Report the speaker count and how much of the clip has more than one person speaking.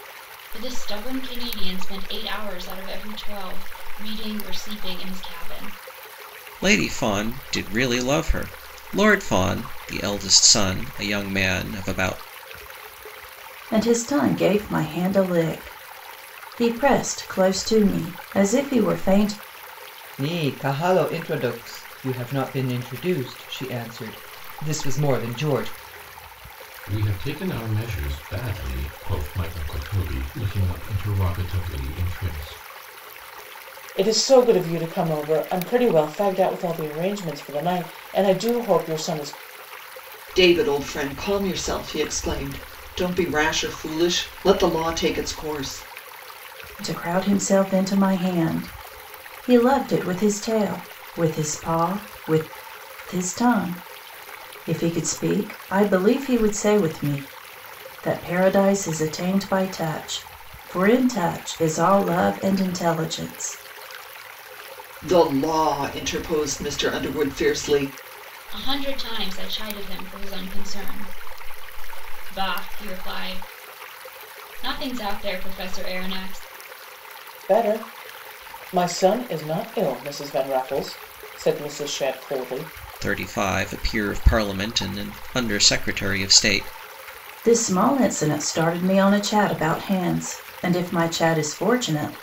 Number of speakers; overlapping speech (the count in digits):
7, no overlap